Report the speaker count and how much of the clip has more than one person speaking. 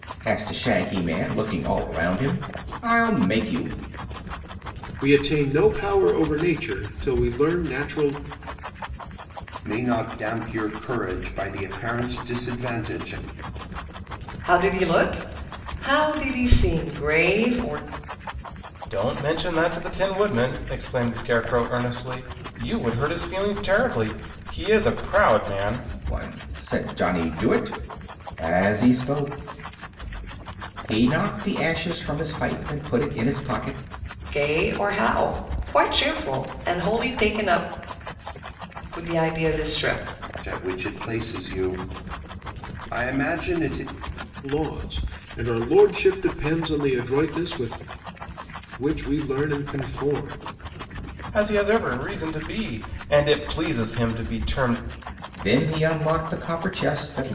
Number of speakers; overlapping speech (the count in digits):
5, no overlap